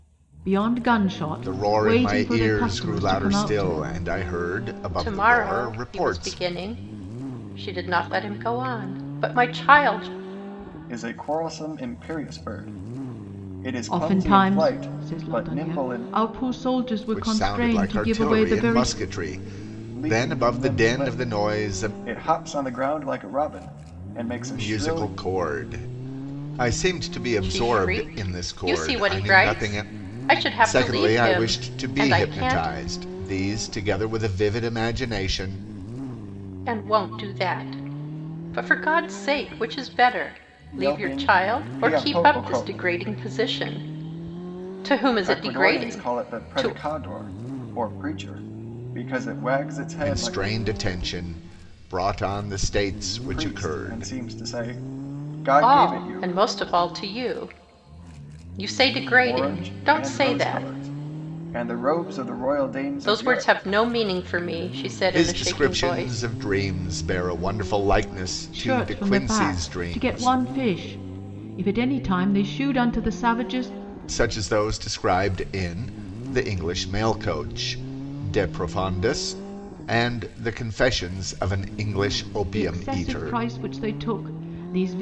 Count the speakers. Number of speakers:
4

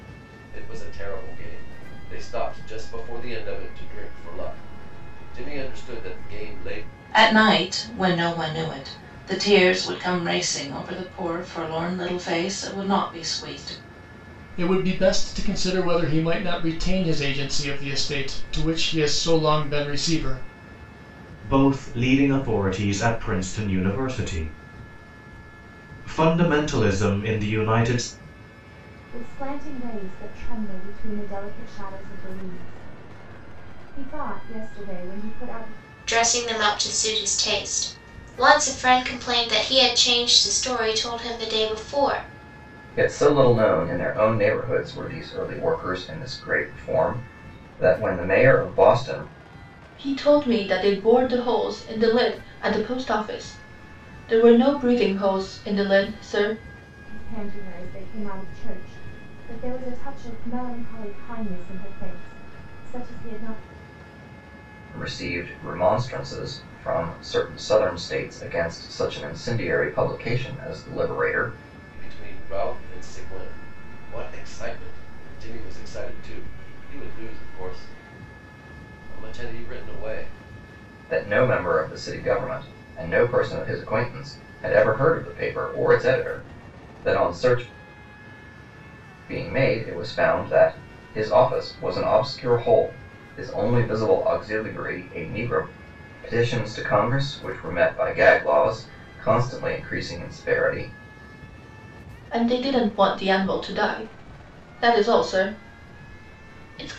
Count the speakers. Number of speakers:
8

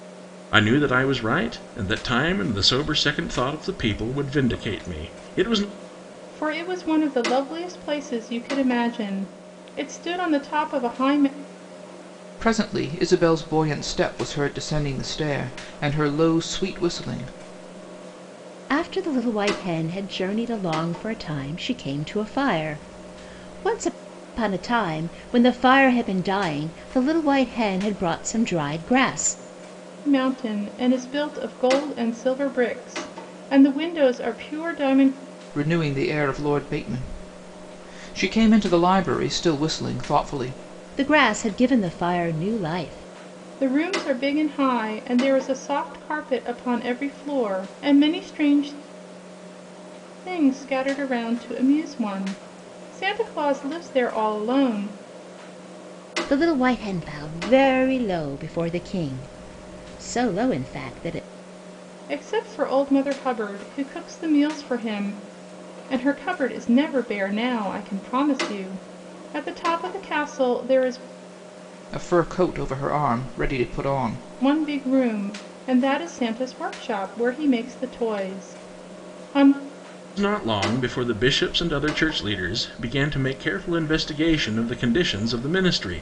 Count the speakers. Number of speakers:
4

